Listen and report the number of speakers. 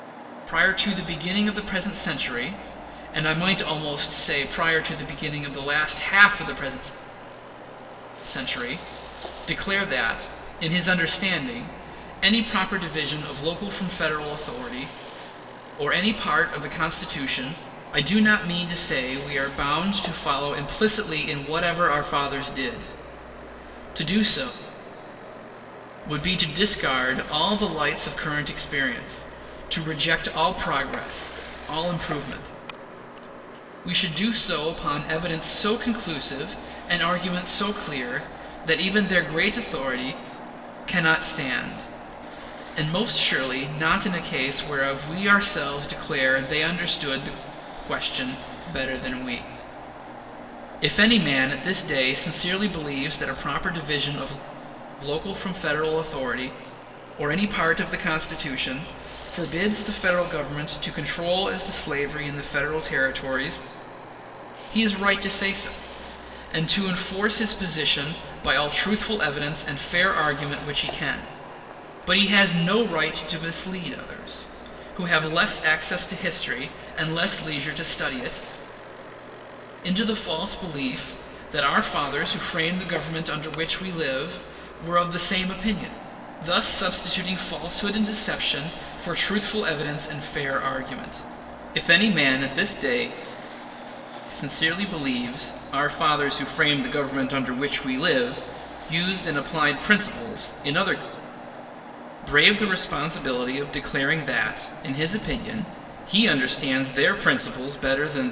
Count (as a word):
one